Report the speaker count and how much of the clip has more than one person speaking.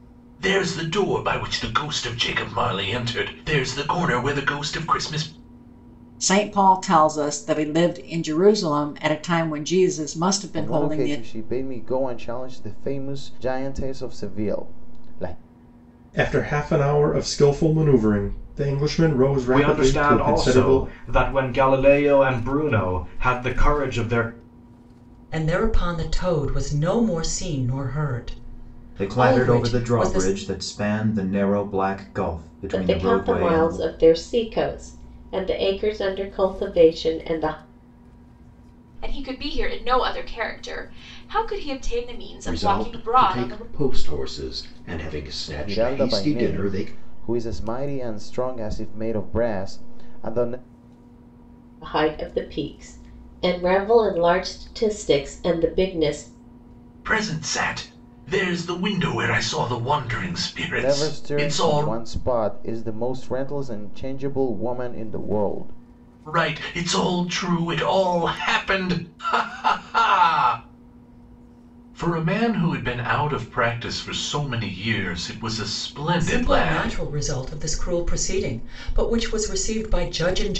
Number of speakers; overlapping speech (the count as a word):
ten, about 11%